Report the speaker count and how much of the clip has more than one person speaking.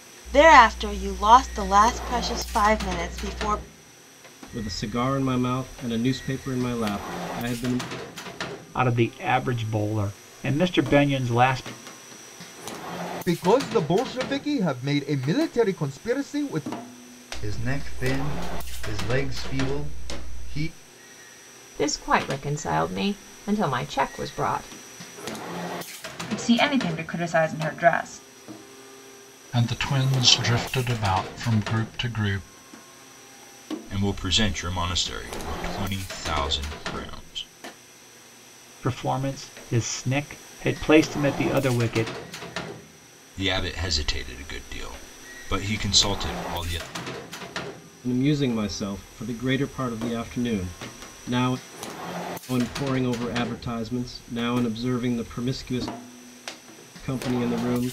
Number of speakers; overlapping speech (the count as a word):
nine, no overlap